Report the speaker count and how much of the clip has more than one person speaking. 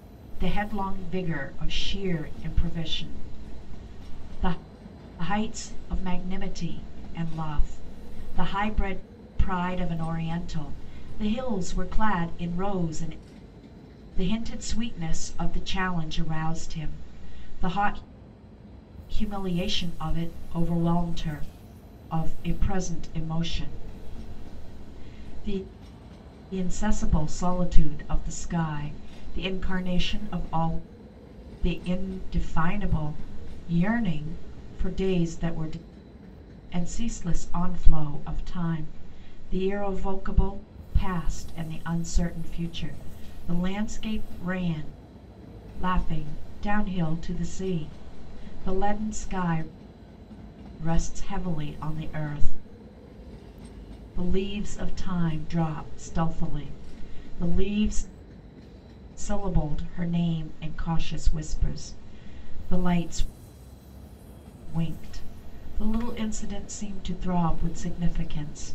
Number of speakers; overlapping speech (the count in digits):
1, no overlap